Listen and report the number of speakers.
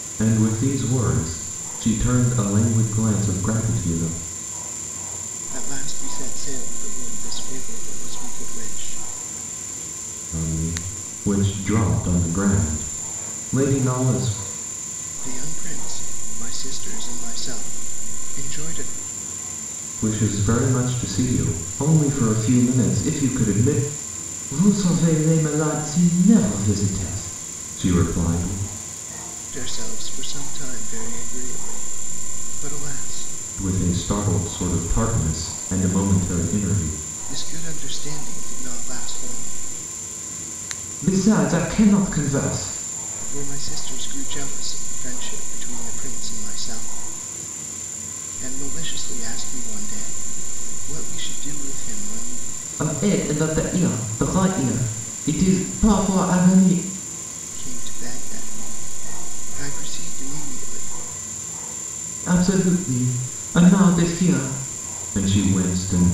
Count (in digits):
2